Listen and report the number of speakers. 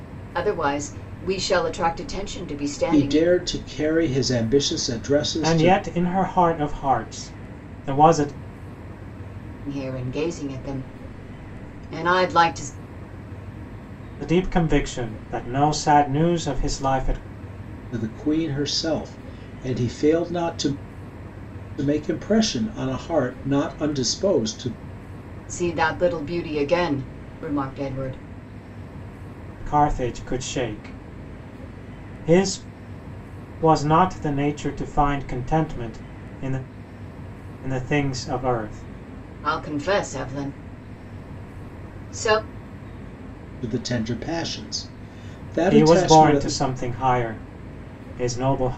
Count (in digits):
3